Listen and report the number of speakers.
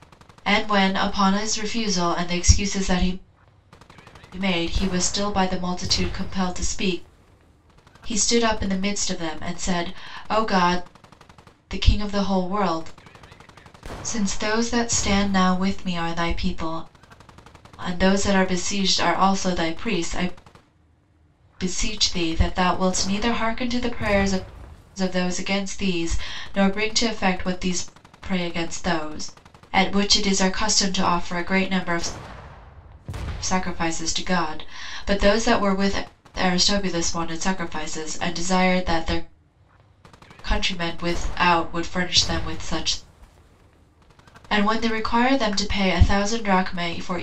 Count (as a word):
one